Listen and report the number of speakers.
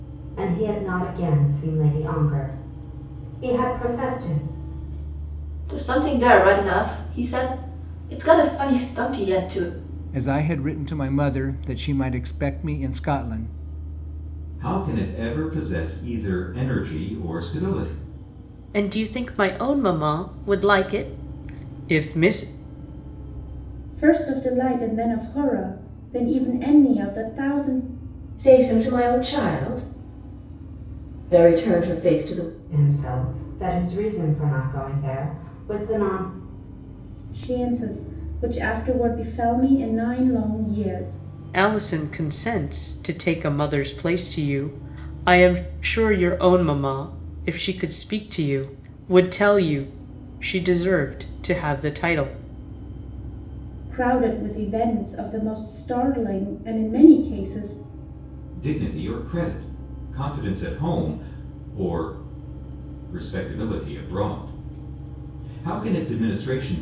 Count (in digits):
7